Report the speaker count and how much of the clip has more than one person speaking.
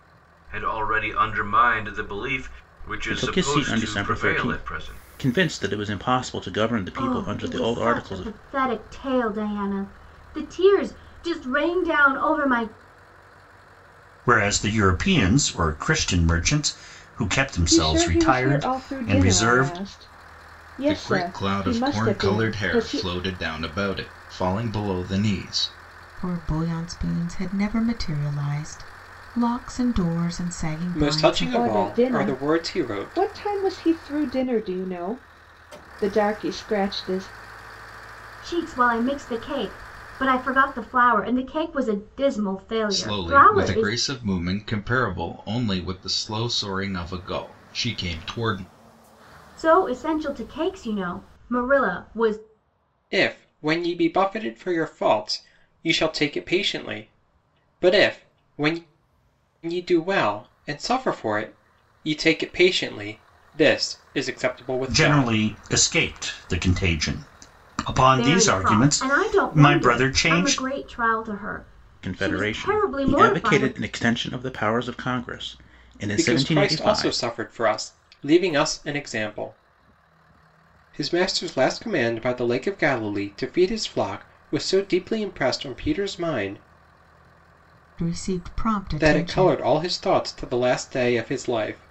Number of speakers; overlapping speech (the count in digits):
8, about 20%